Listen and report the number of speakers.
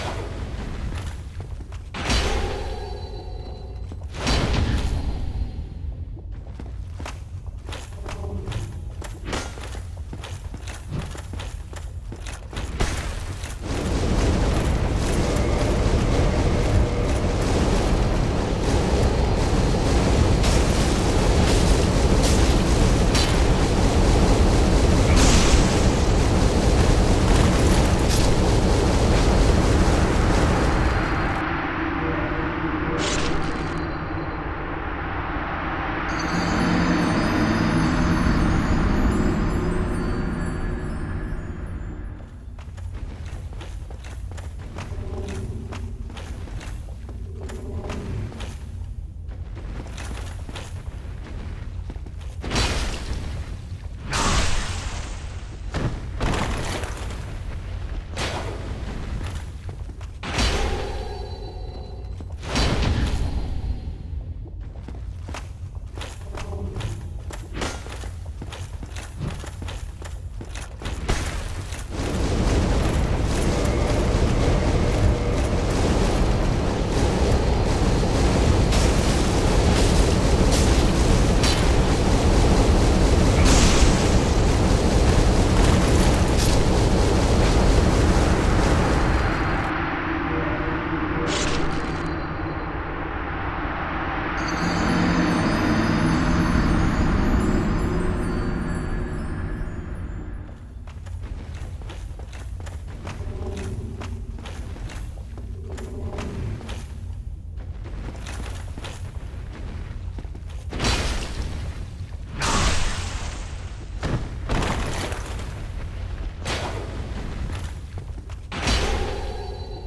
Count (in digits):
0